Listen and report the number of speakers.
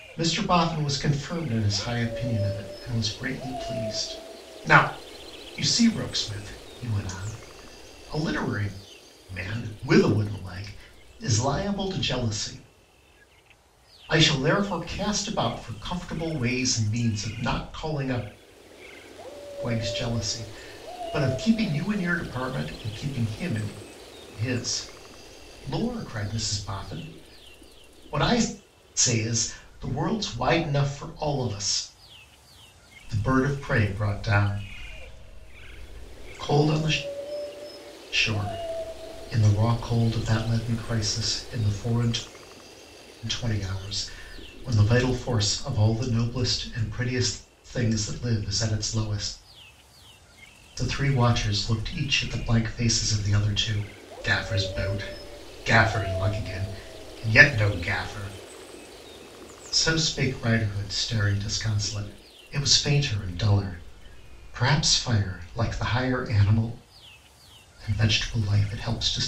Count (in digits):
1